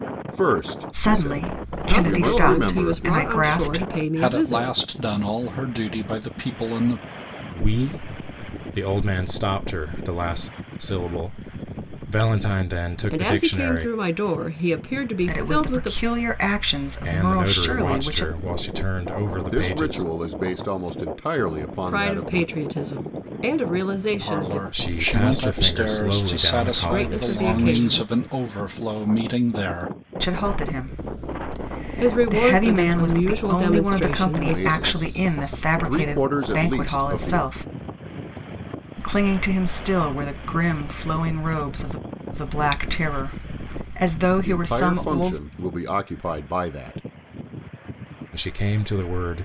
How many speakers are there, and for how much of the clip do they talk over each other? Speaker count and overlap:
five, about 37%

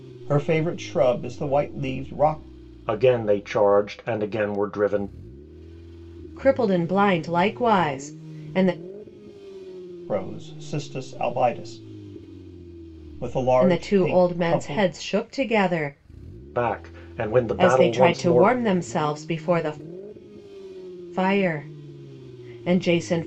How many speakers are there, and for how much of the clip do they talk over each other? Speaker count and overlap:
three, about 10%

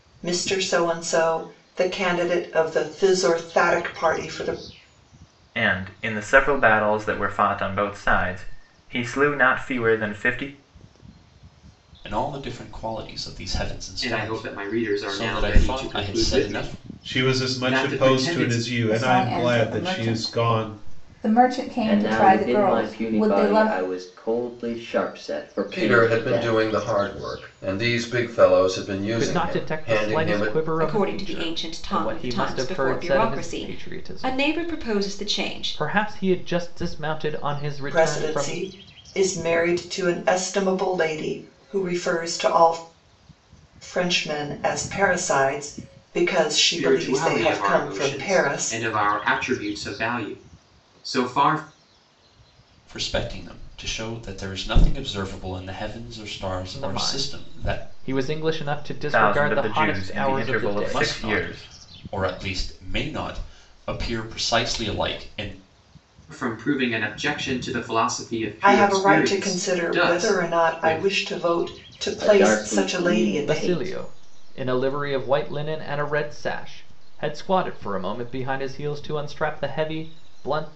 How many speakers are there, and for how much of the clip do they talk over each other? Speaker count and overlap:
ten, about 33%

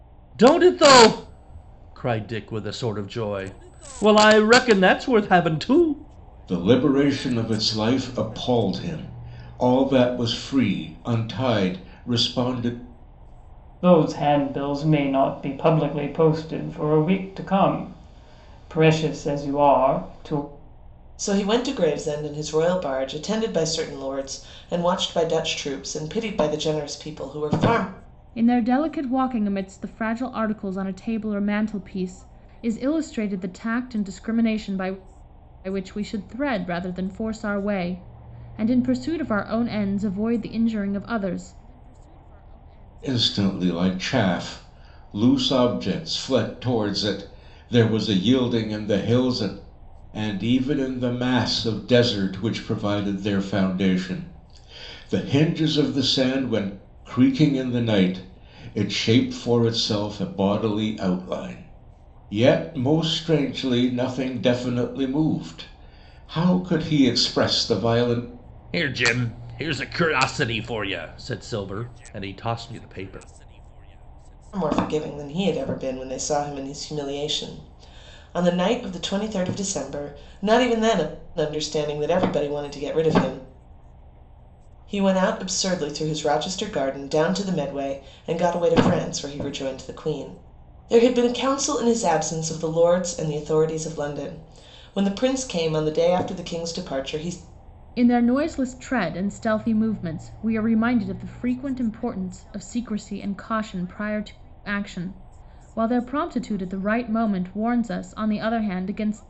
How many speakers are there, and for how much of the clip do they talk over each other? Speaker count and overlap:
five, no overlap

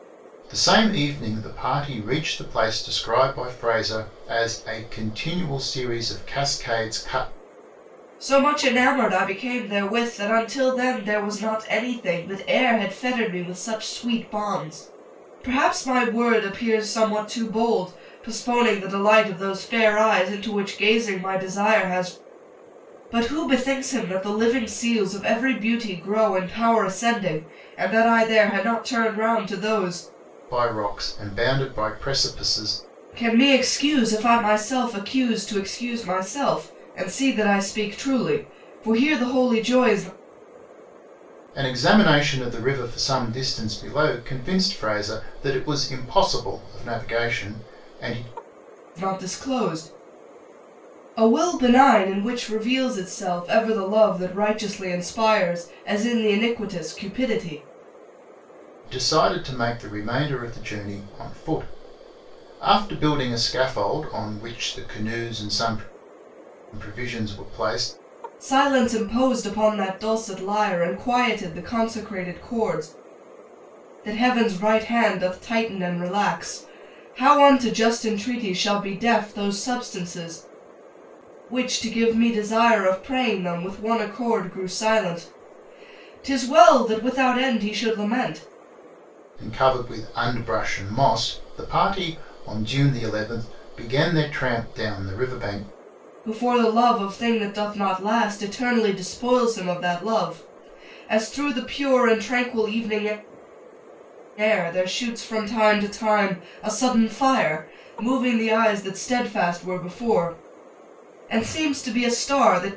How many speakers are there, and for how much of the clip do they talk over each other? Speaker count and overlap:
two, no overlap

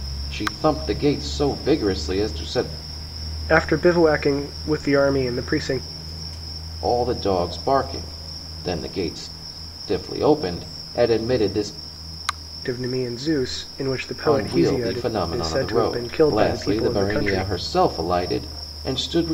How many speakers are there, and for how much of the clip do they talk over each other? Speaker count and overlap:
two, about 15%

